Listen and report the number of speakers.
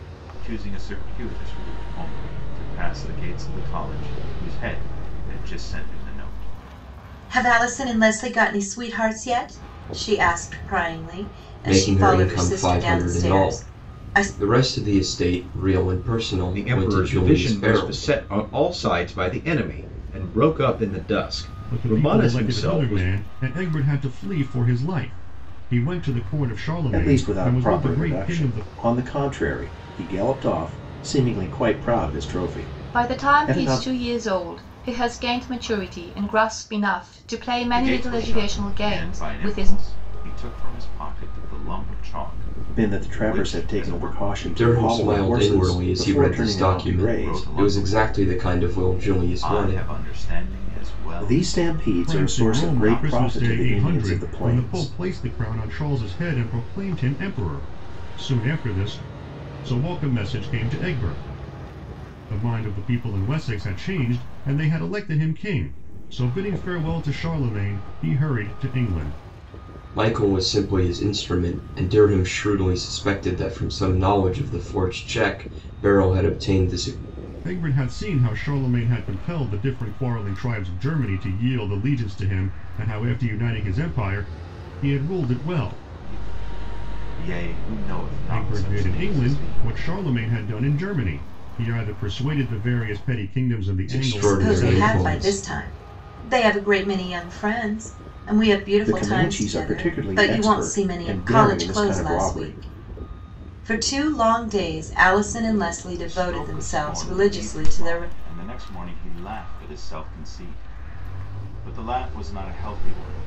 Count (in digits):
7